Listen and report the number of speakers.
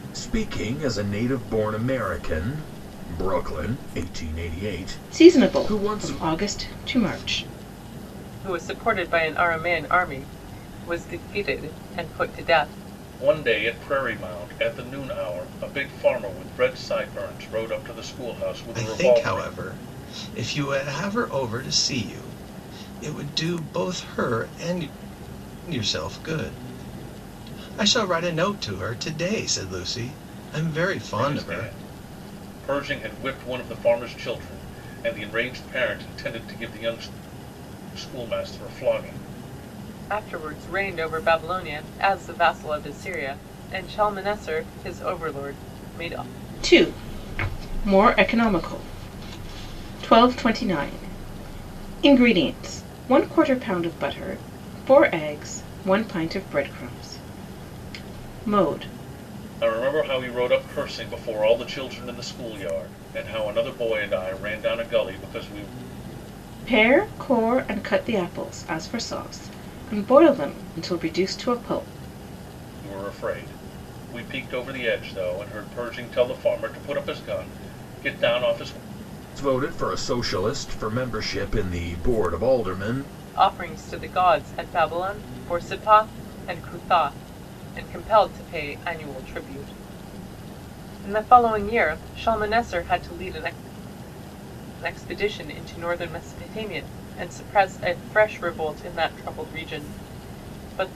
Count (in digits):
5